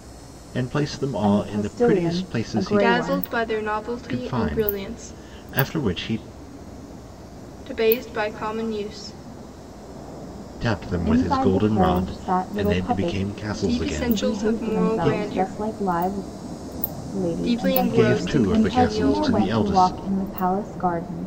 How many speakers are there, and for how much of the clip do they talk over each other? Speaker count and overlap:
3, about 48%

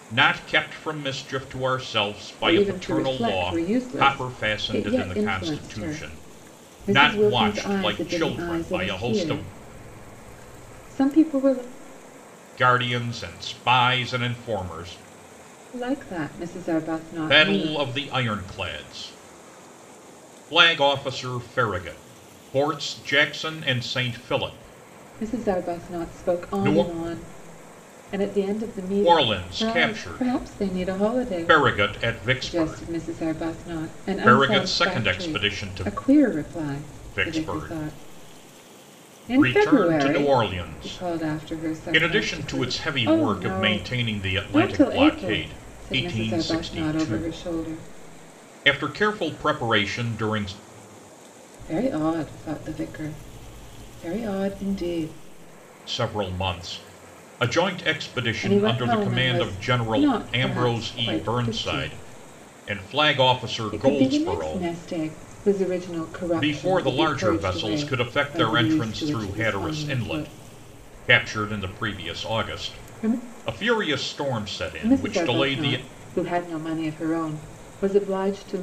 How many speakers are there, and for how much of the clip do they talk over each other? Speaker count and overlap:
2, about 43%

